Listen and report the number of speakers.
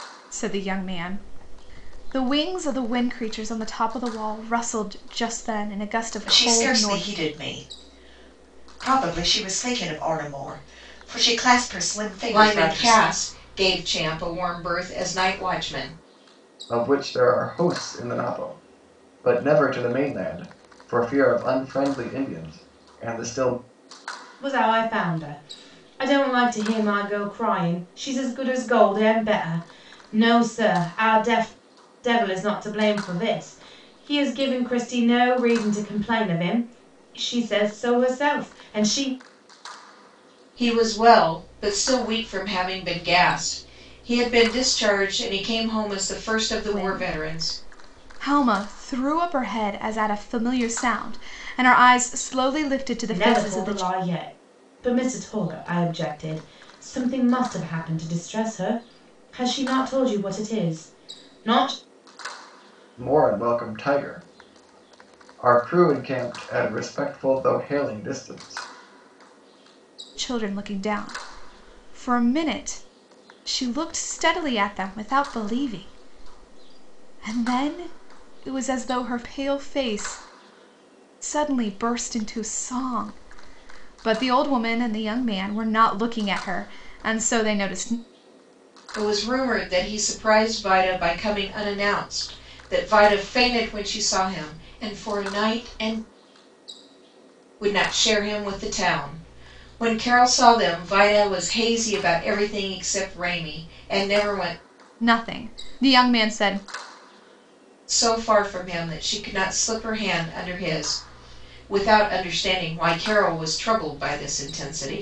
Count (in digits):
5